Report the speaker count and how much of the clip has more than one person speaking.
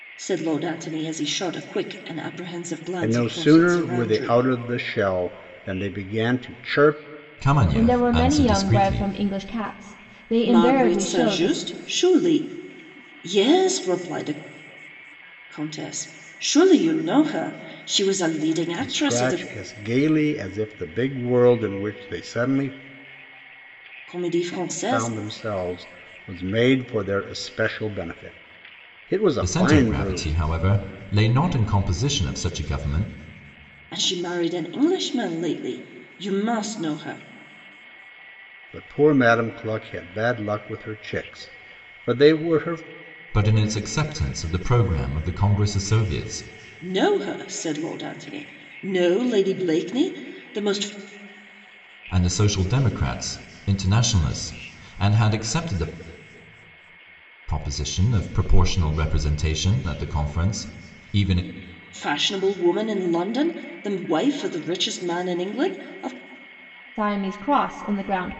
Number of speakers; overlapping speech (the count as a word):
four, about 9%